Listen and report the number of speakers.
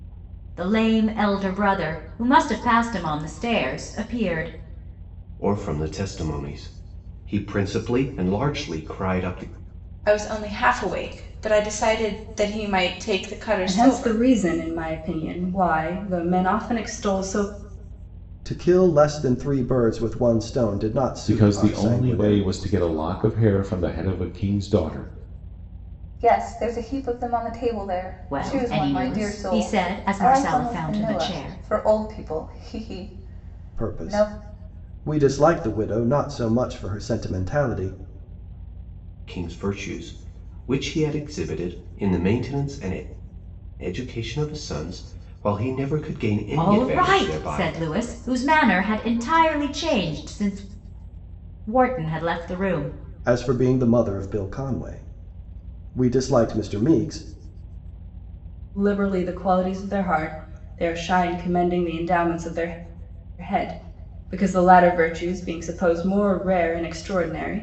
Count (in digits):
7